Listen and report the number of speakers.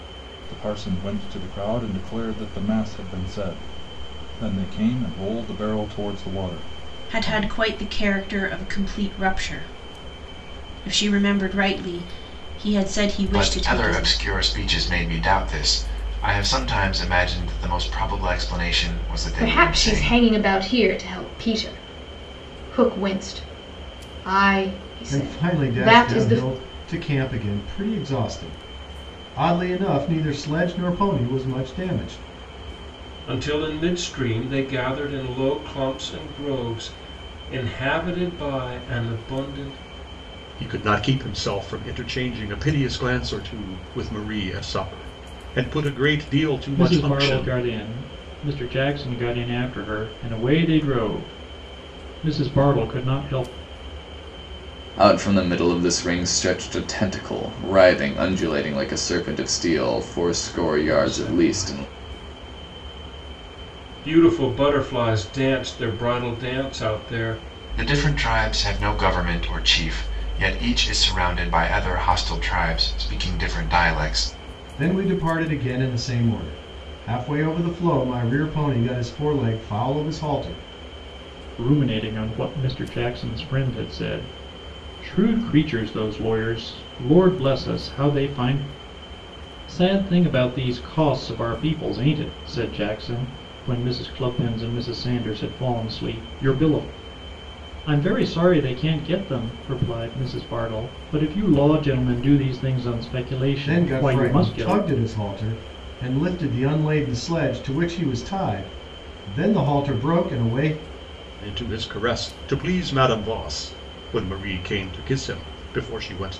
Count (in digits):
9